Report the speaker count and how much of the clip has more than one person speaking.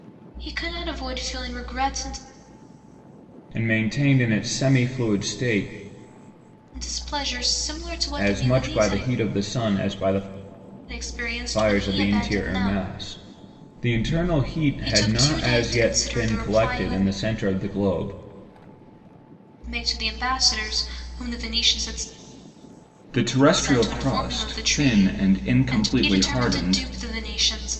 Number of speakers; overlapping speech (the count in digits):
2, about 28%